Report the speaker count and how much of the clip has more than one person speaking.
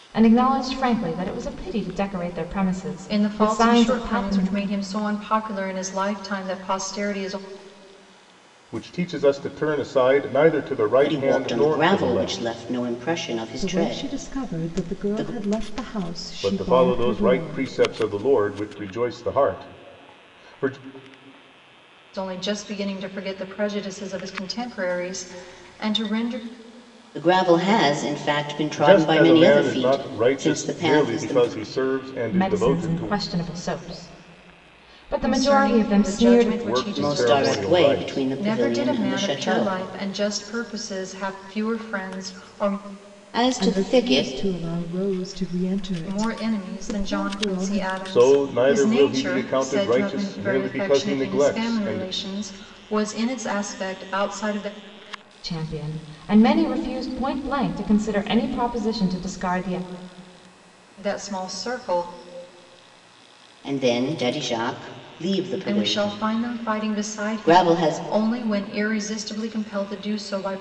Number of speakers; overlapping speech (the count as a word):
five, about 33%